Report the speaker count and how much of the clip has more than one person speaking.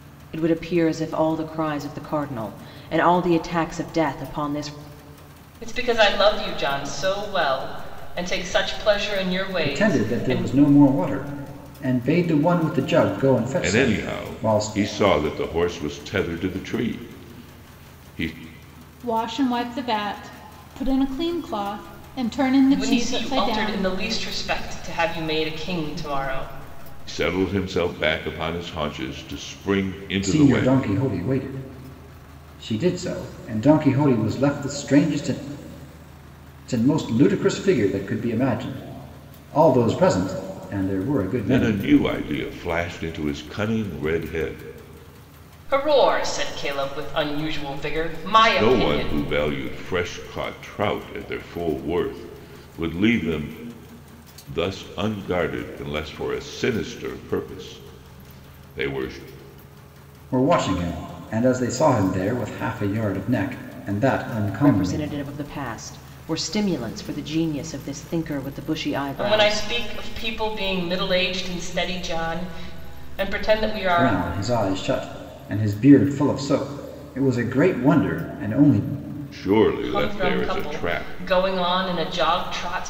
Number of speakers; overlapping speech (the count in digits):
5, about 9%